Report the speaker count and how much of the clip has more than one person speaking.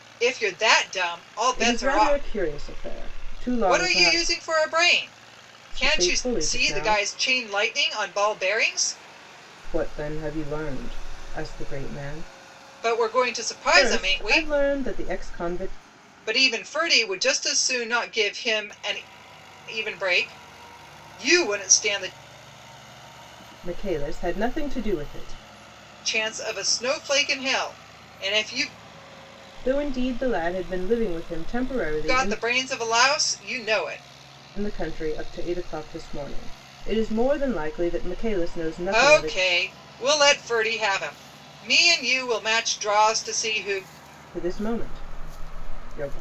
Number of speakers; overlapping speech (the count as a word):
two, about 9%